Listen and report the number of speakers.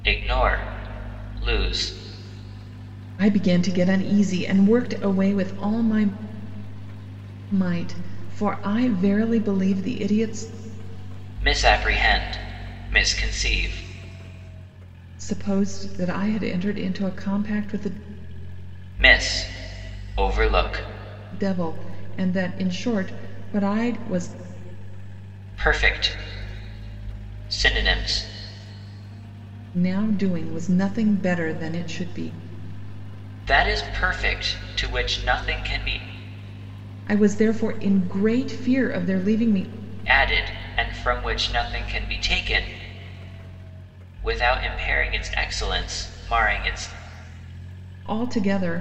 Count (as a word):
two